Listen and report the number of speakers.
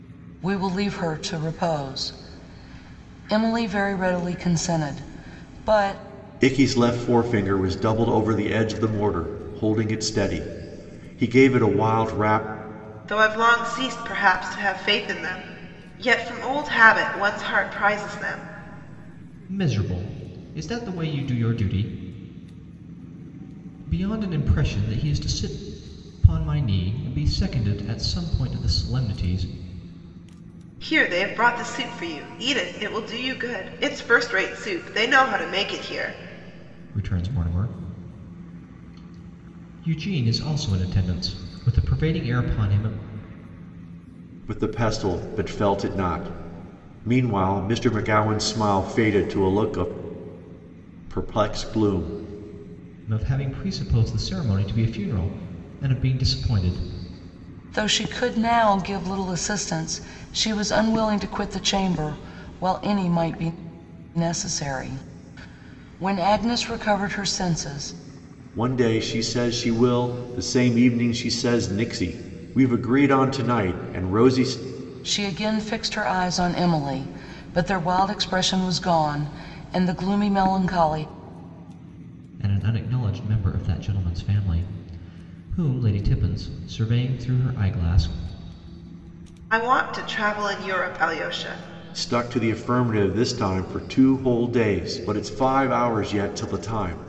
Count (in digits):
4